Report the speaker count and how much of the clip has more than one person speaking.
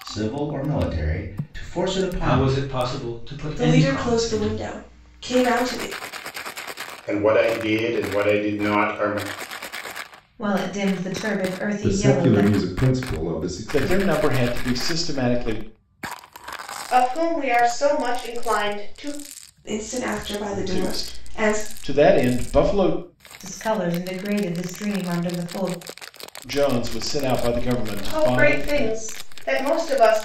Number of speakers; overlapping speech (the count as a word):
eight, about 15%